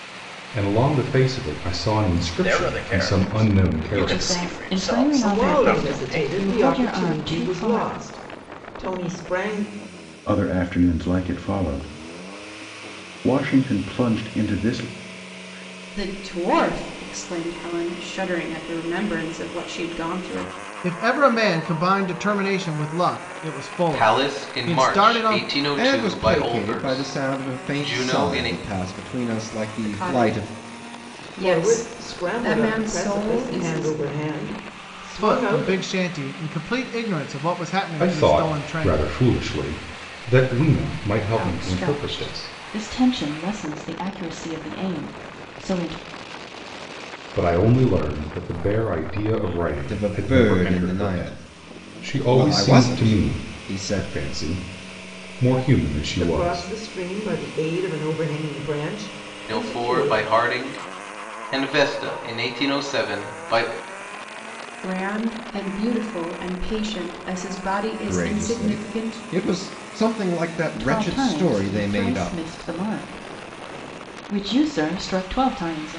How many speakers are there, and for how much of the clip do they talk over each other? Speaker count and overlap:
9, about 32%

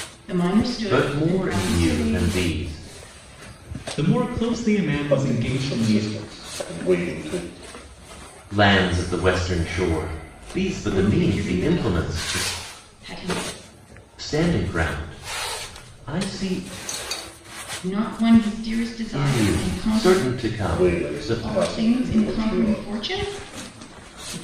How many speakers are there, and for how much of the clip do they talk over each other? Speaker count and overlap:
4, about 32%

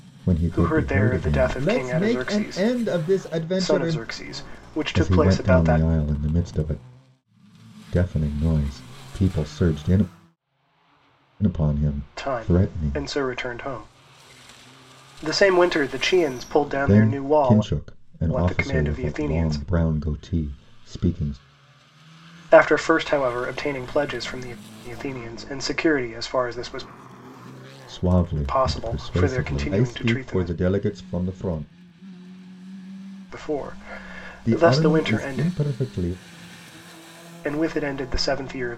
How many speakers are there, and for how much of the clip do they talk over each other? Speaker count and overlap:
2, about 26%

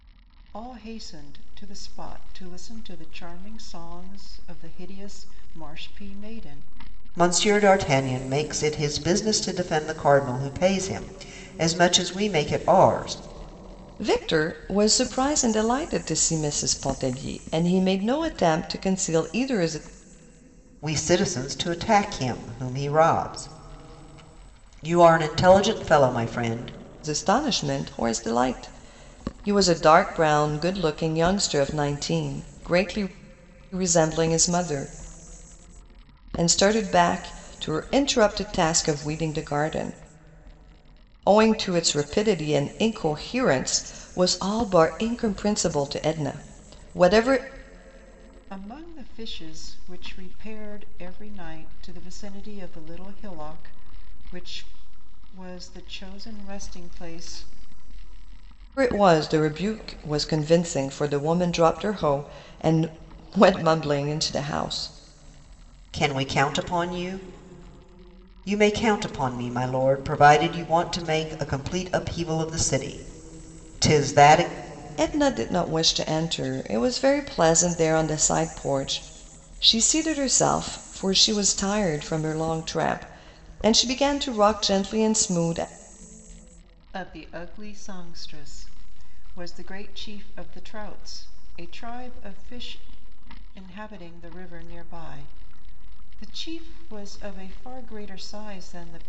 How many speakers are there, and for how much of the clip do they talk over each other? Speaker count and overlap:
3, no overlap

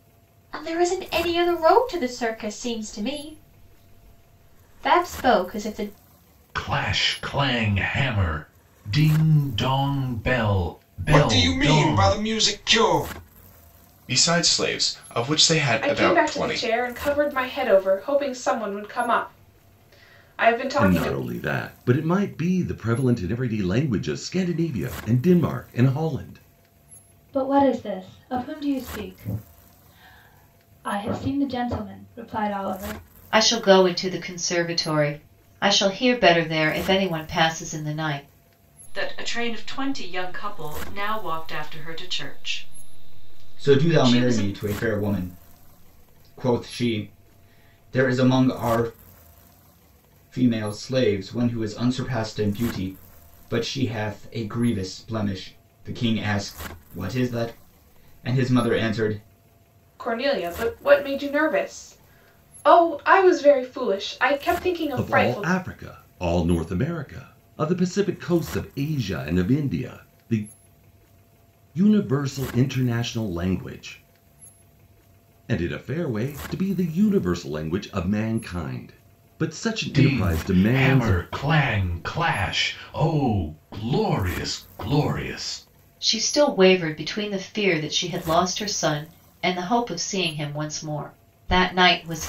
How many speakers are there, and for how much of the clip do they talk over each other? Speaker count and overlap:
10, about 6%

